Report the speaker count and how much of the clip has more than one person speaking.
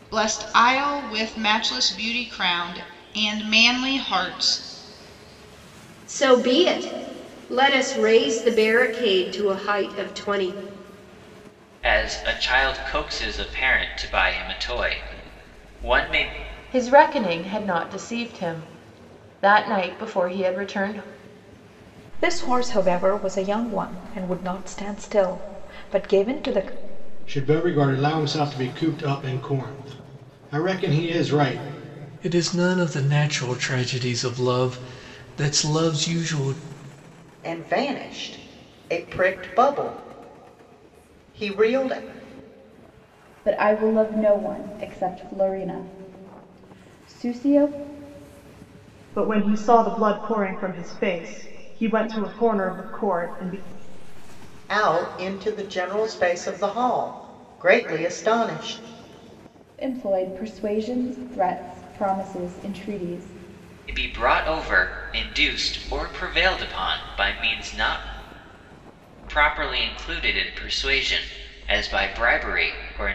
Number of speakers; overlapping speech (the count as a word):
ten, no overlap